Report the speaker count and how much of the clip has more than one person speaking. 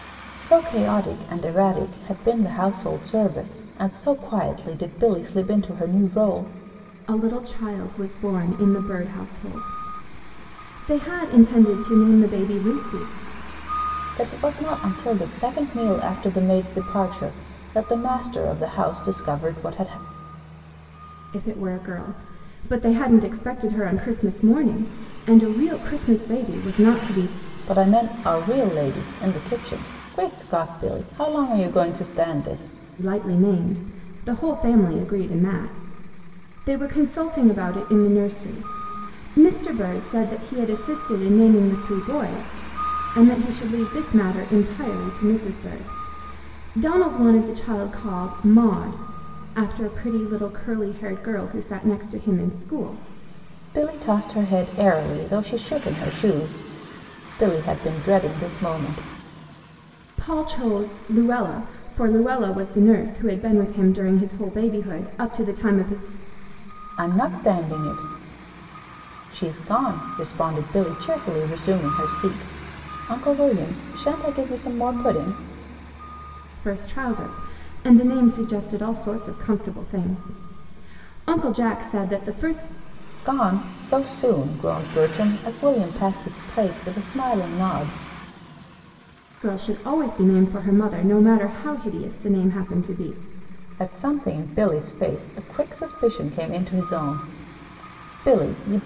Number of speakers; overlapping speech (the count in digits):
2, no overlap